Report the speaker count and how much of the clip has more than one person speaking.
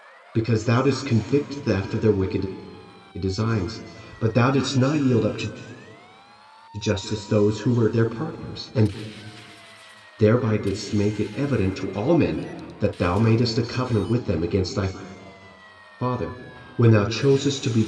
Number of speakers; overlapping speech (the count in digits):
1, no overlap